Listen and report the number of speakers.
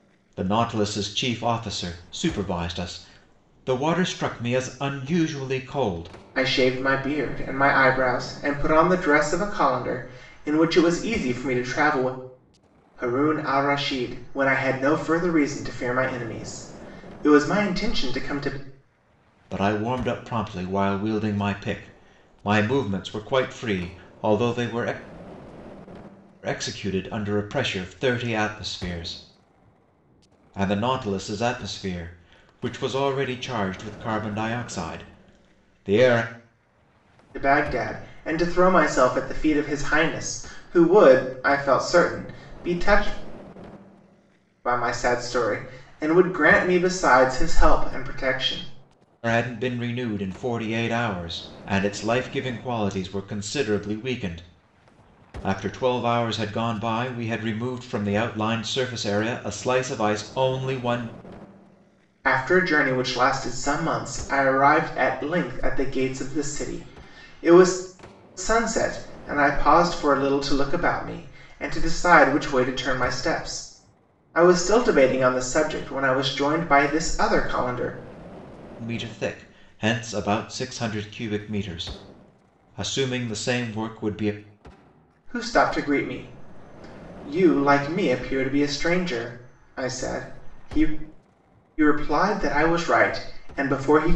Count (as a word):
two